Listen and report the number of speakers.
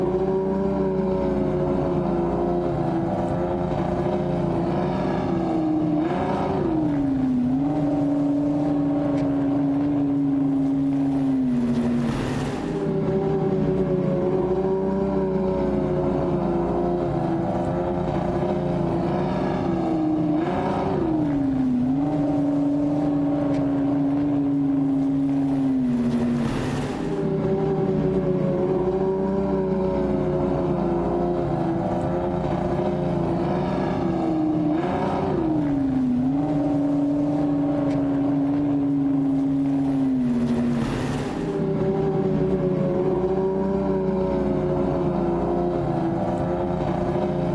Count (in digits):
0